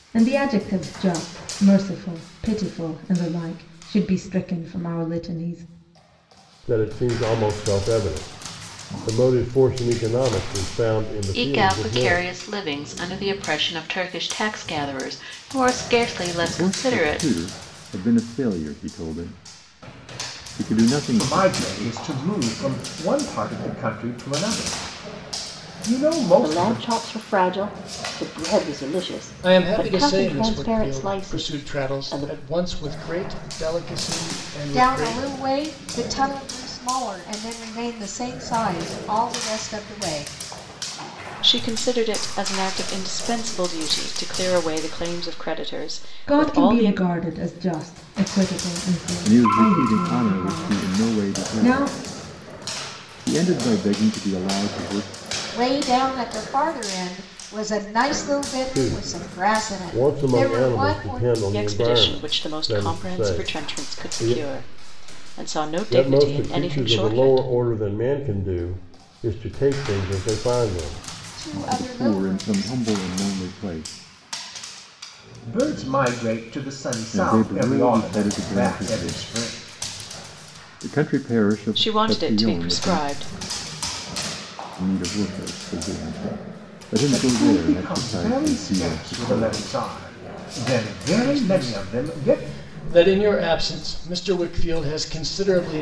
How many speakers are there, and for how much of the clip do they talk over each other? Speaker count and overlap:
9, about 28%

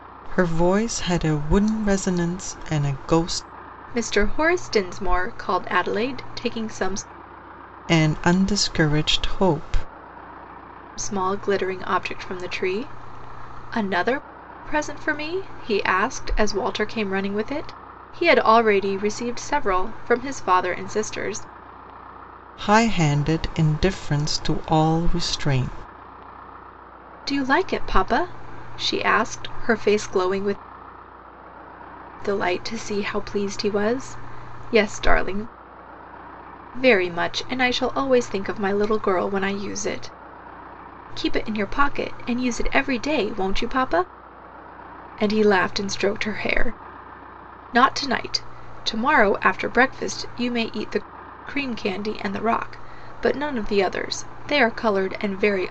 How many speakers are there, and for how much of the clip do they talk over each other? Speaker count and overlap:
2, no overlap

